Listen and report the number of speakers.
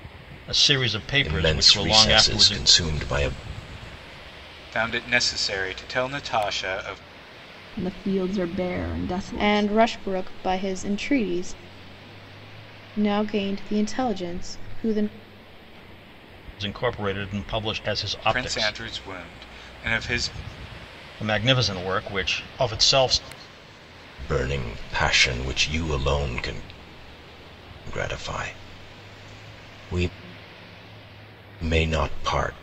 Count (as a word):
five